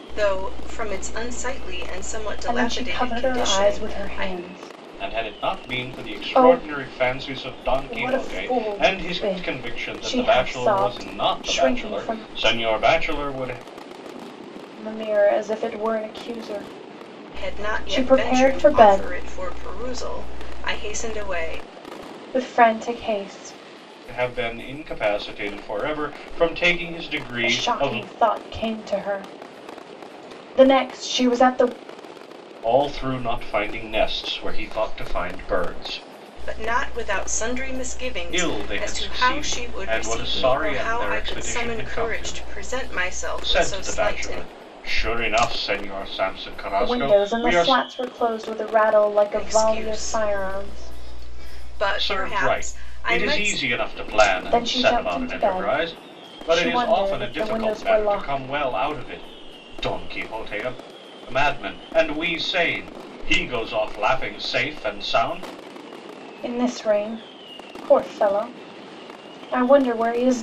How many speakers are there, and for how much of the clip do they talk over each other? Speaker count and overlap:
three, about 33%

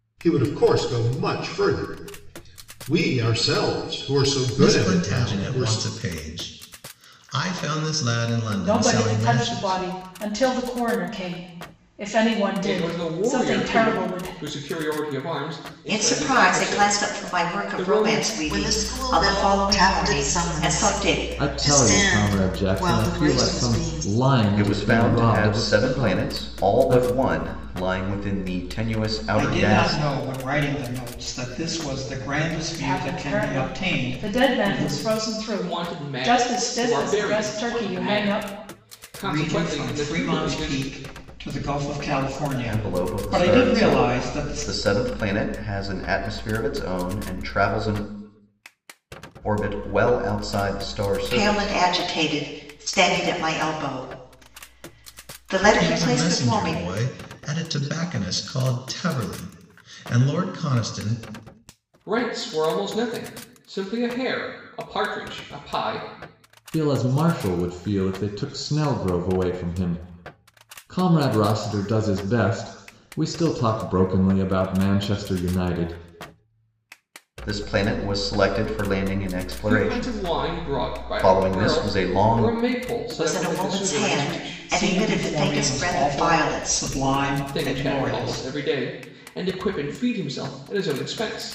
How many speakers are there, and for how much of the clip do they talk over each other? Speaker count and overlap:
nine, about 37%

